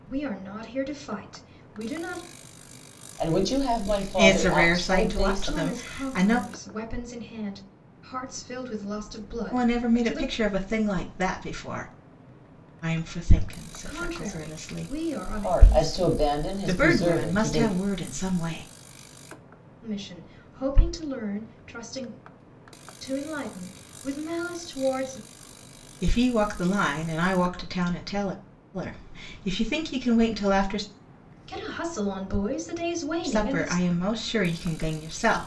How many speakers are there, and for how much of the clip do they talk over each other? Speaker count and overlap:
three, about 19%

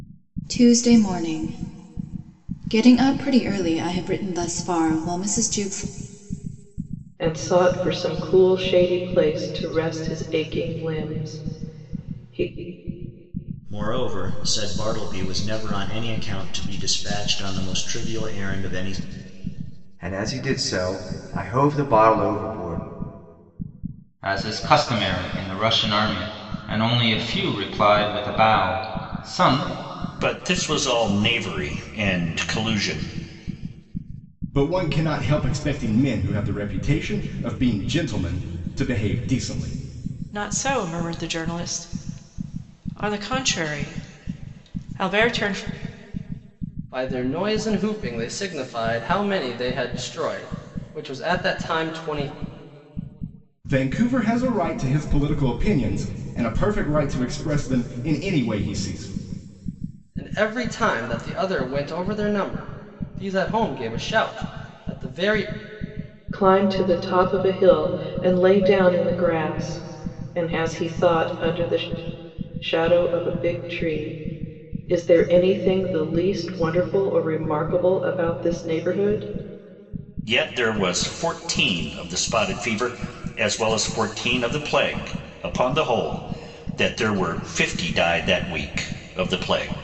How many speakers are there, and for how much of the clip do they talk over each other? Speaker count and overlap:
nine, no overlap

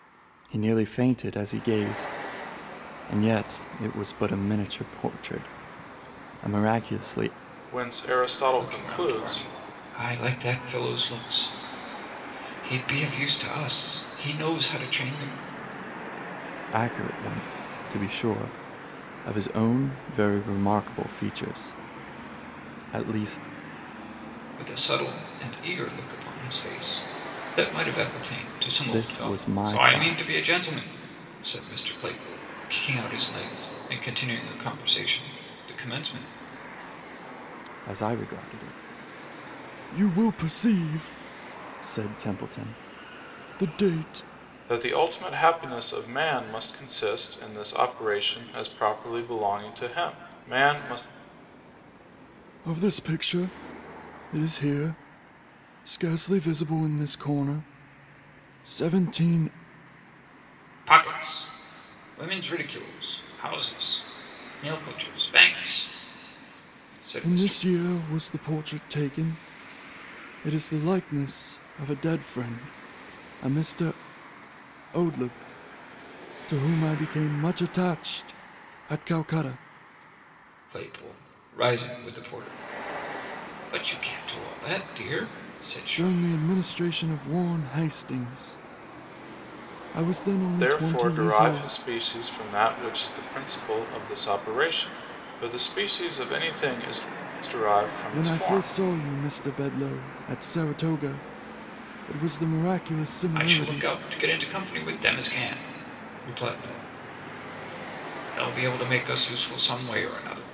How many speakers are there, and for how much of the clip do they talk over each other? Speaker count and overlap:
three, about 5%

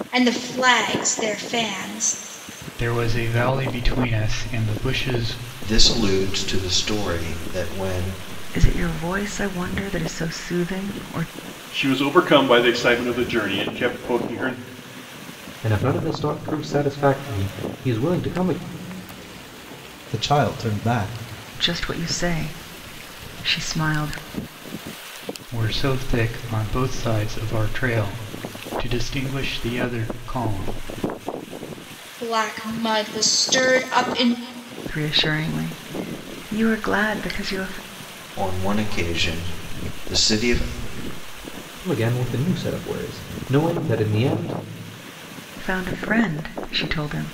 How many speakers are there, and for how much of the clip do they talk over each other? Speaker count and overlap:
seven, no overlap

